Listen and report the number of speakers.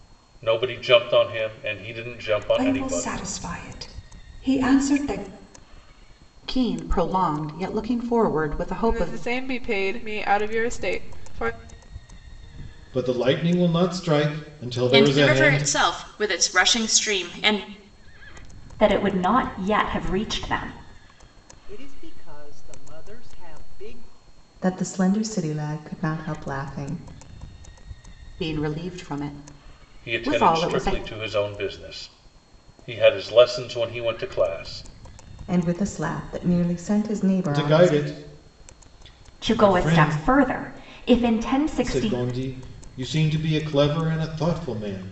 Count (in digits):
9